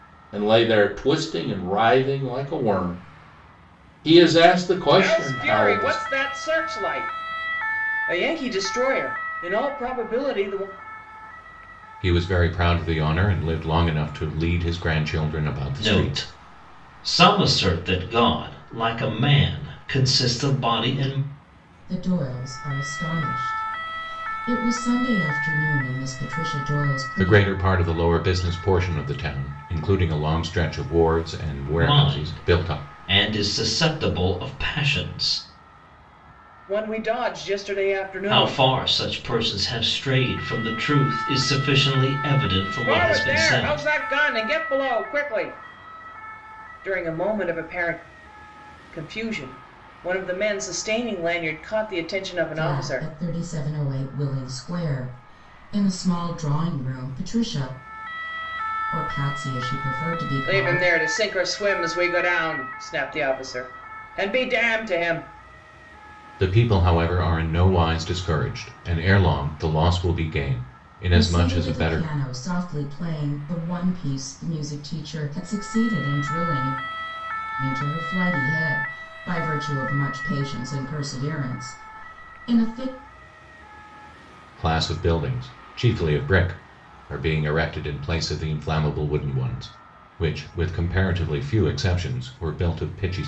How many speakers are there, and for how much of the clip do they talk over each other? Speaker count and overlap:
5, about 7%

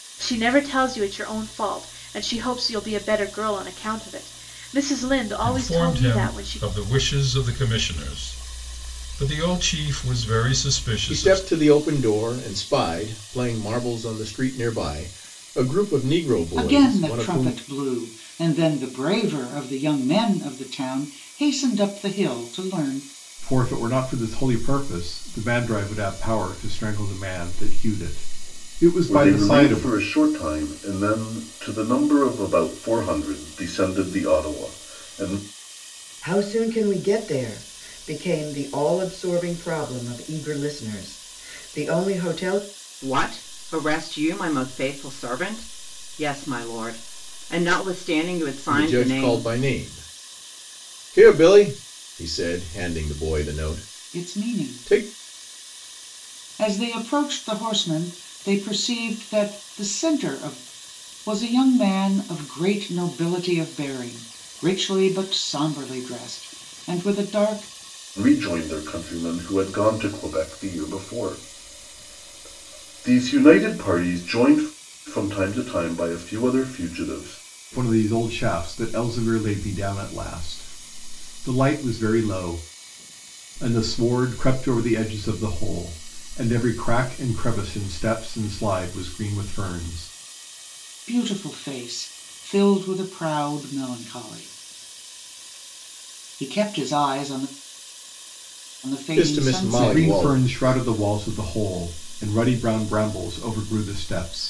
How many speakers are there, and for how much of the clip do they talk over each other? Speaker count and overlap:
8, about 7%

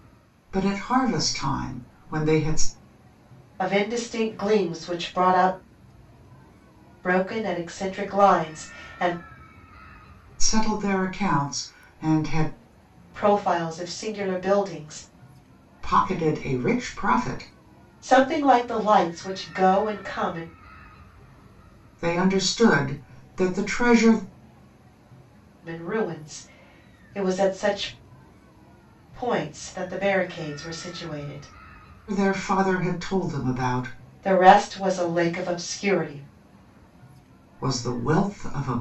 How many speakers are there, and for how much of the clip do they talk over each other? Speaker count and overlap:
2, no overlap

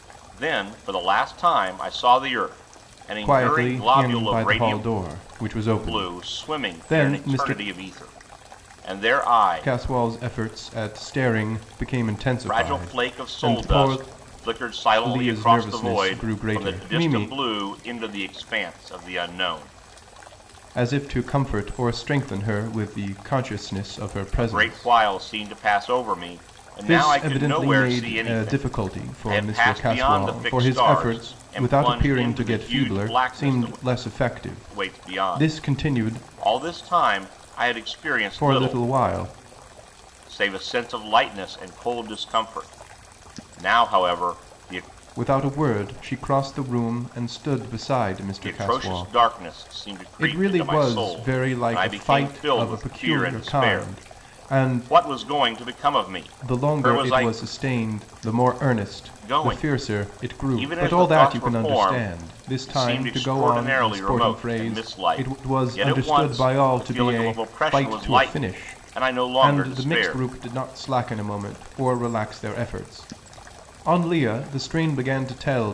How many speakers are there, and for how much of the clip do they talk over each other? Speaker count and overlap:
2, about 44%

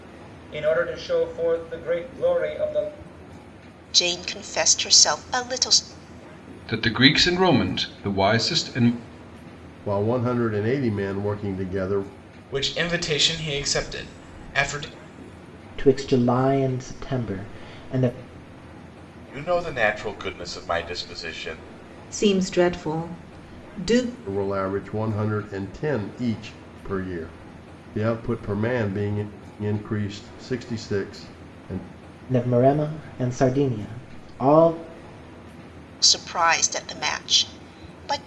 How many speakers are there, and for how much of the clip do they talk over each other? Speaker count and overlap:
8, no overlap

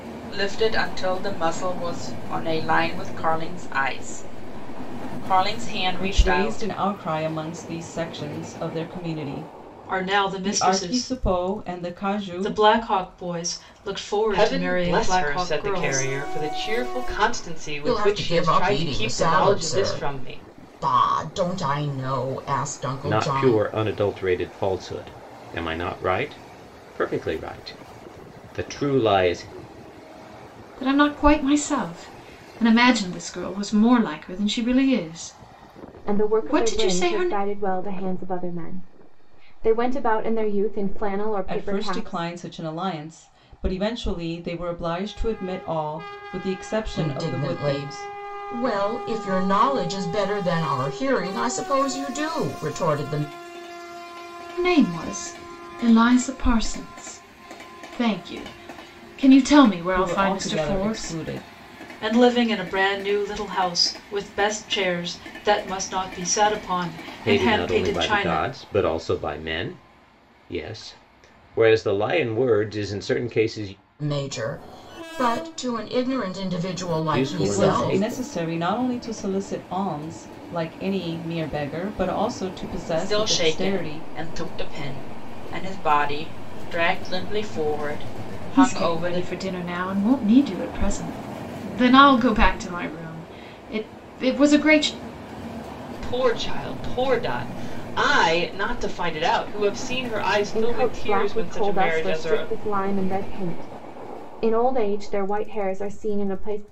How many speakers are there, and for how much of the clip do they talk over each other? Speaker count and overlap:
8, about 18%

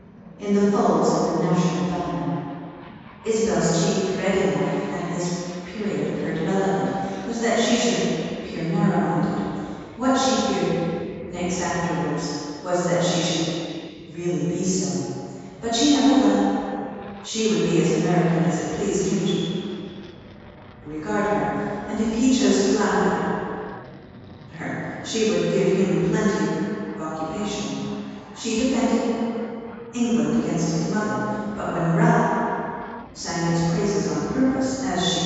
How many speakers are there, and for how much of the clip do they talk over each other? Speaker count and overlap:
1, no overlap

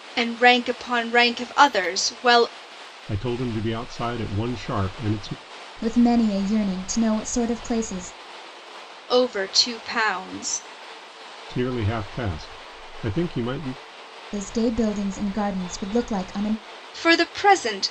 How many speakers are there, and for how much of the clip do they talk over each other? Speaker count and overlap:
3, no overlap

